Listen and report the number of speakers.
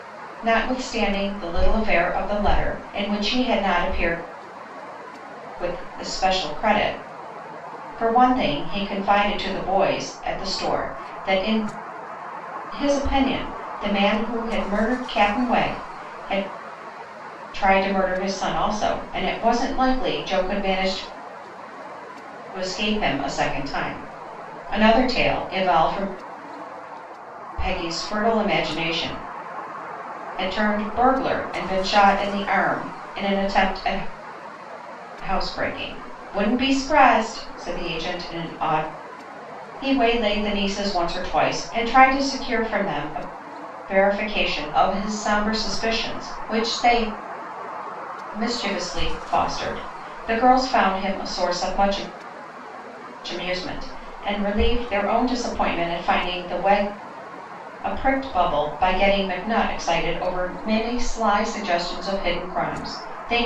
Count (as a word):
one